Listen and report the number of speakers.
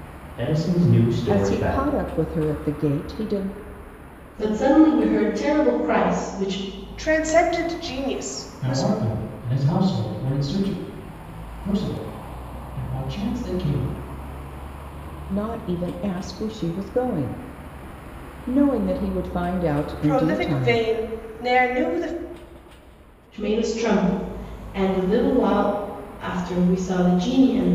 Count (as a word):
five